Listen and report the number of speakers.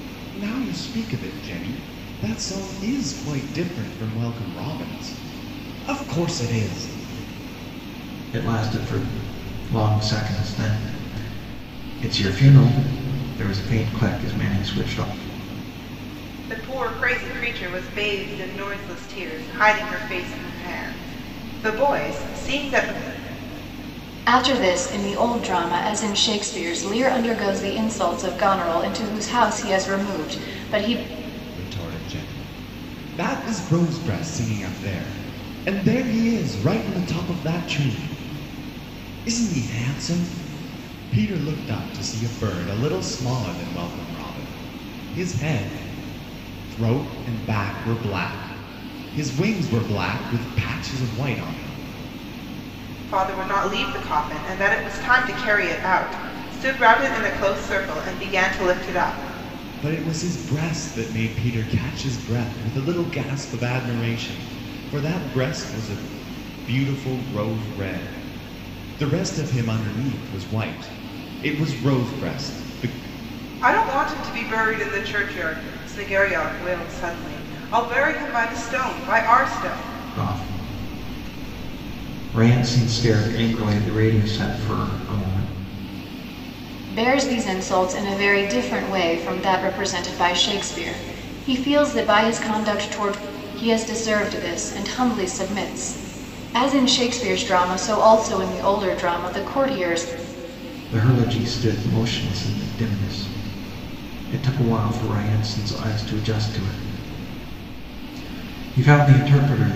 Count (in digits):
4